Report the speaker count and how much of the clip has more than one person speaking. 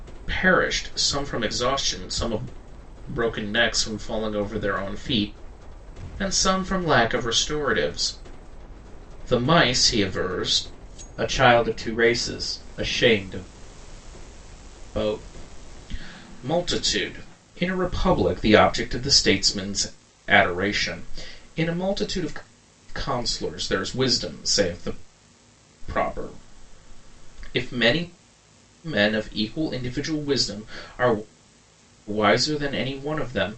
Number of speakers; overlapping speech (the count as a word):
one, no overlap